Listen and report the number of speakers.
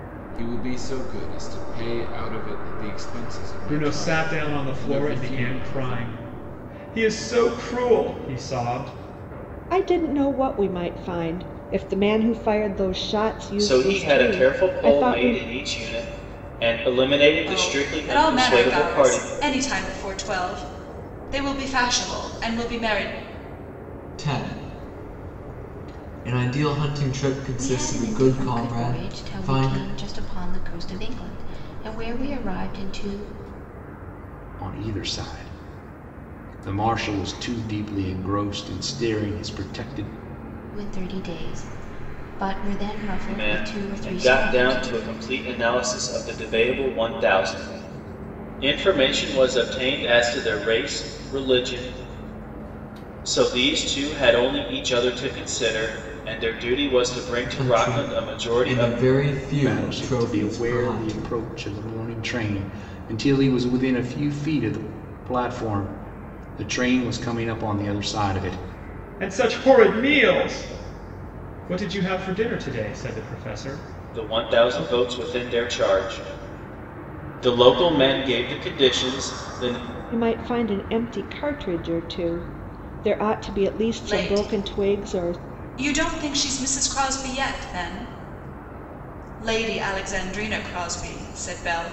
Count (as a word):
eight